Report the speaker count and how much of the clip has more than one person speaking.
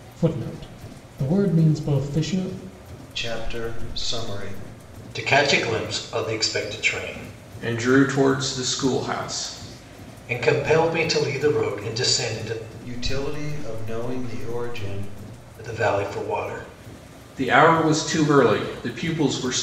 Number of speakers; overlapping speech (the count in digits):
4, no overlap